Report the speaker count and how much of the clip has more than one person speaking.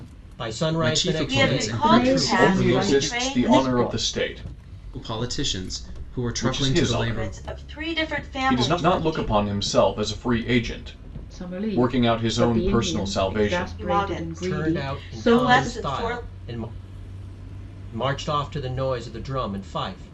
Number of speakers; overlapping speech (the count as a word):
five, about 54%